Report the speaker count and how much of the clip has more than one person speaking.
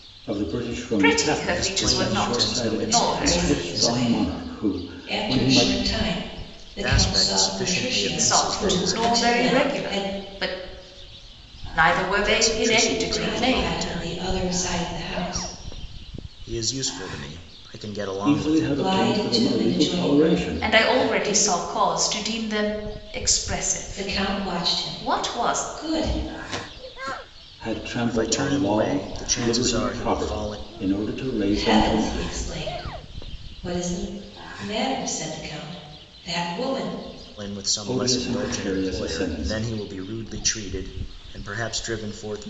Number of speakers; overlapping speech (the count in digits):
4, about 45%